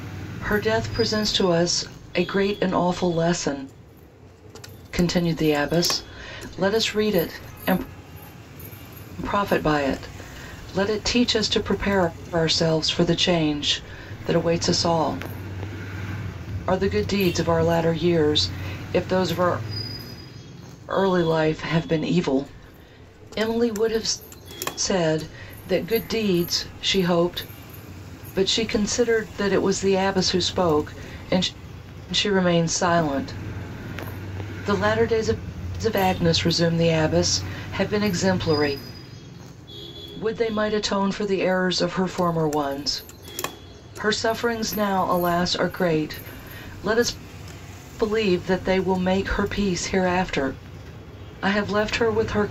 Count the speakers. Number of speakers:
one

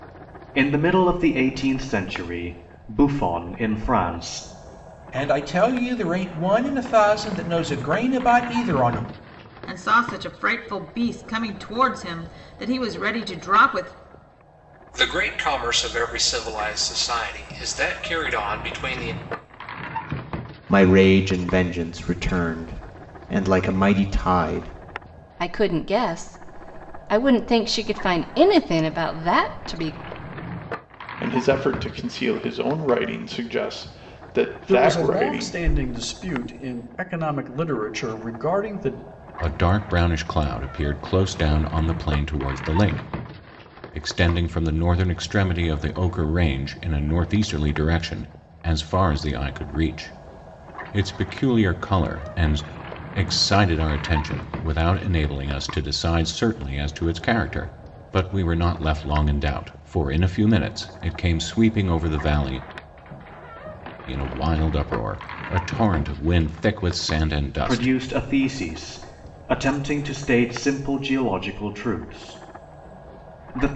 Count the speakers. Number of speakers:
nine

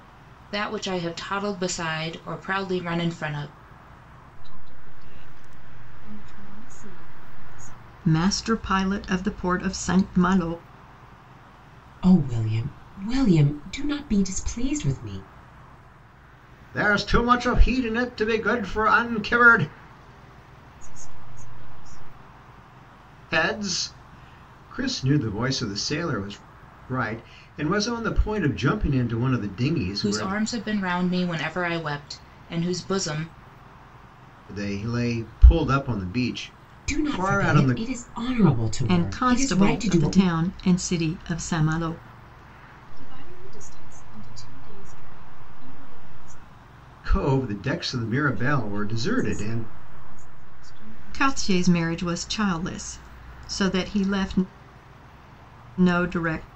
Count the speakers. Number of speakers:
five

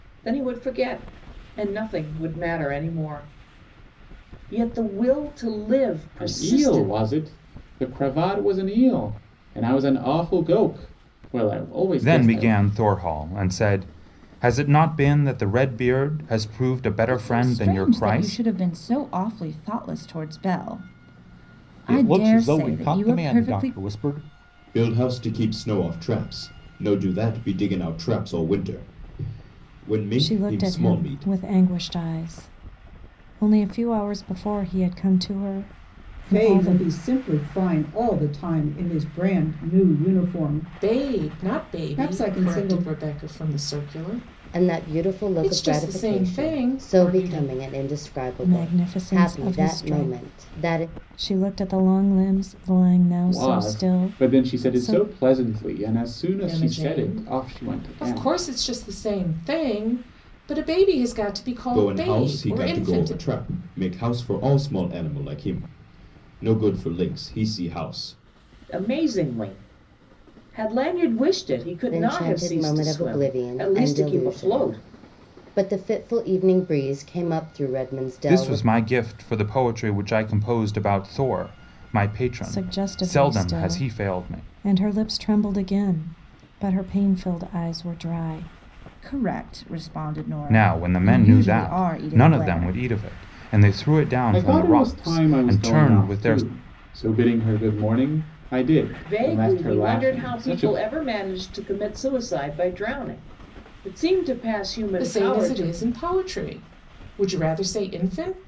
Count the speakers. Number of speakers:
ten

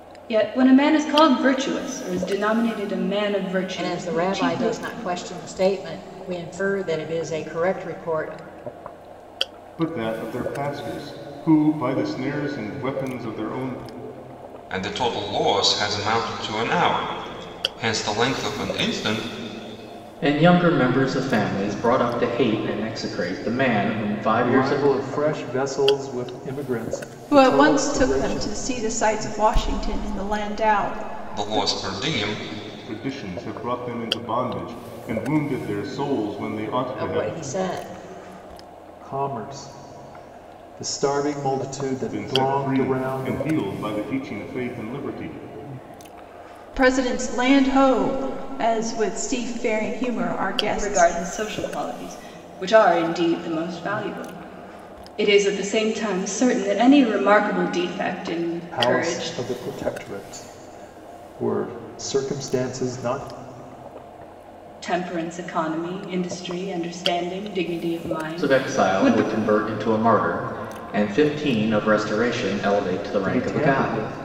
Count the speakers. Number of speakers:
seven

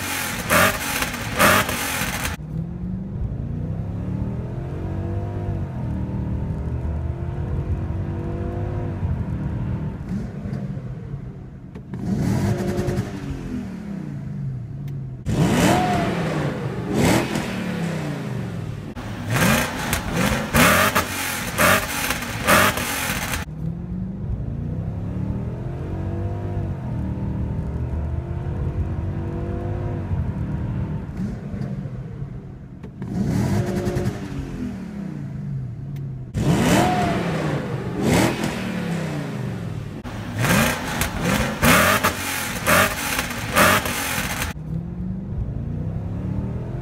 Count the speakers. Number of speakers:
zero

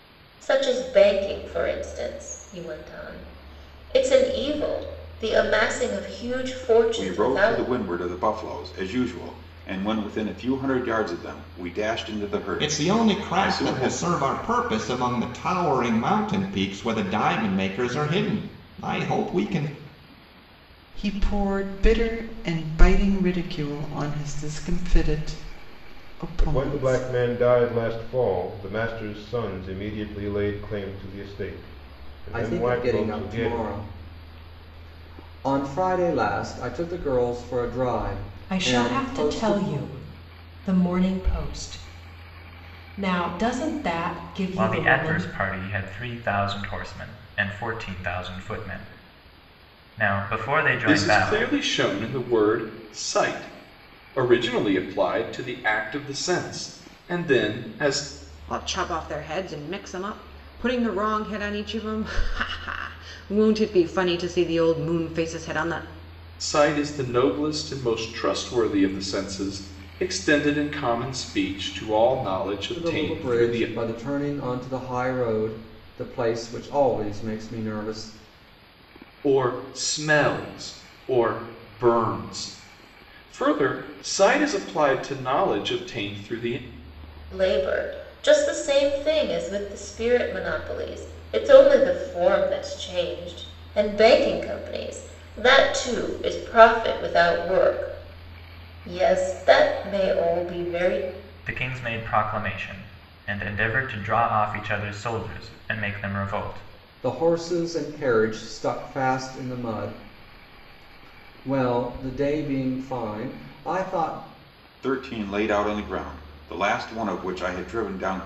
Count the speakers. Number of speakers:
ten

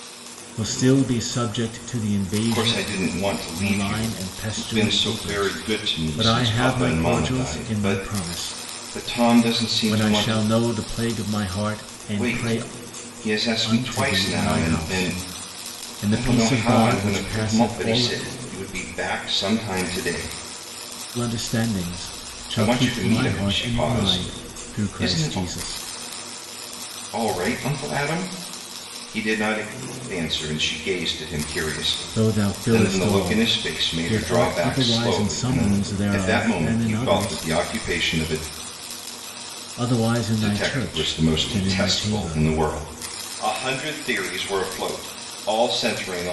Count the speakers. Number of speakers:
two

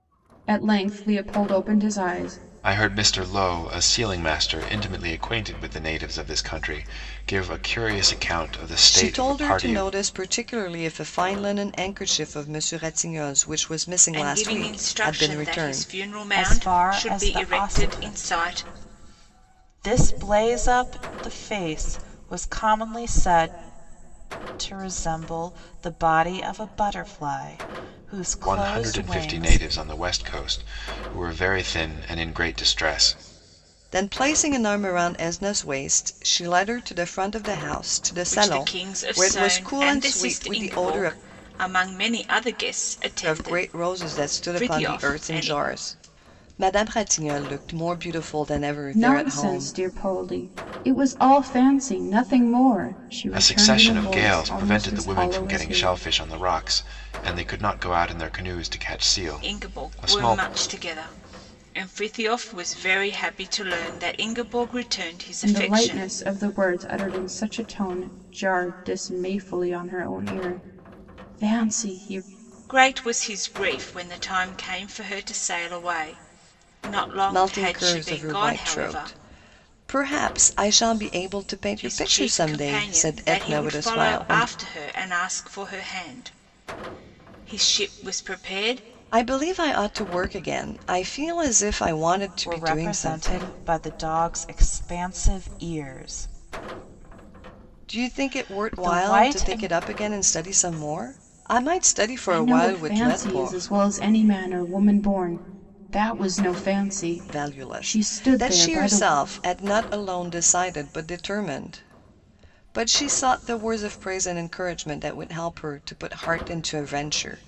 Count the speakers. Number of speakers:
five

